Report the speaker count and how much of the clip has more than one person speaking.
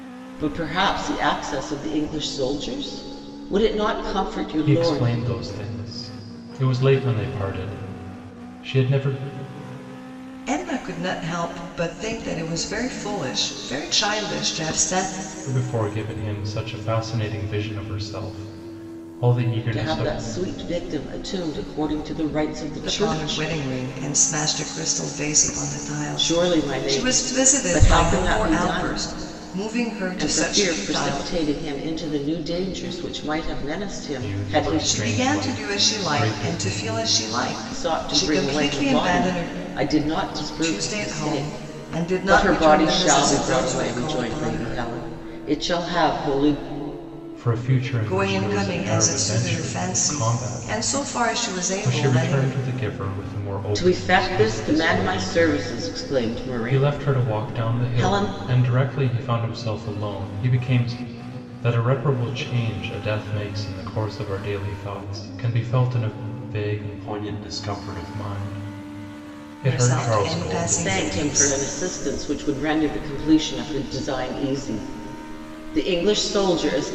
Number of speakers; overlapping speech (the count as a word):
three, about 31%